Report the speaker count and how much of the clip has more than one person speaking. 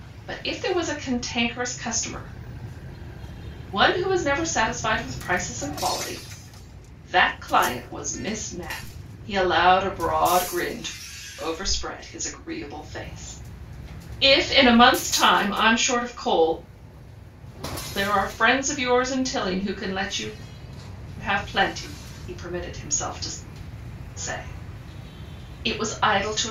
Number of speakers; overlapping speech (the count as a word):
one, no overlap